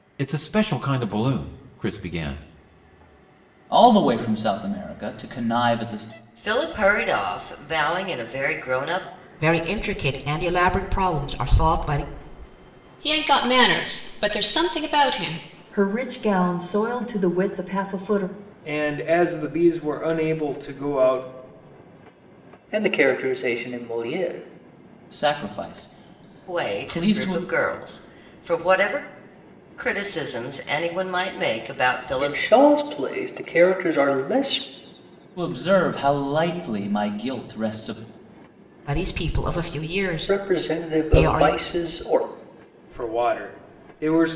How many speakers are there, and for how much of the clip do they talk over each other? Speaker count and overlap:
8, about 6%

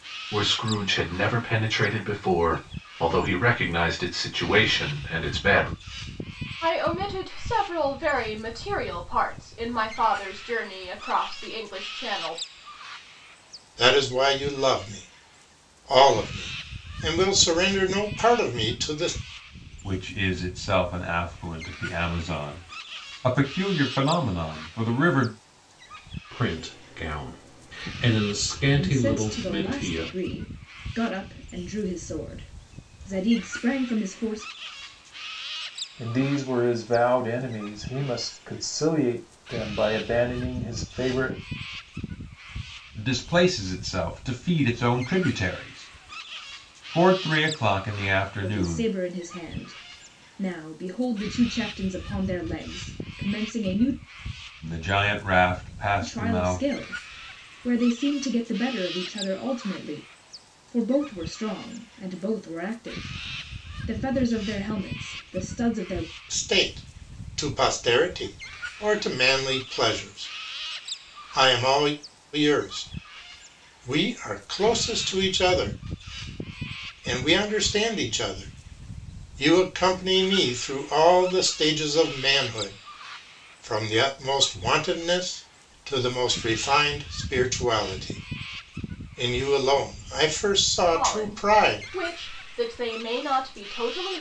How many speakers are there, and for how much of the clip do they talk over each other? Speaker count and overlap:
7, about 4%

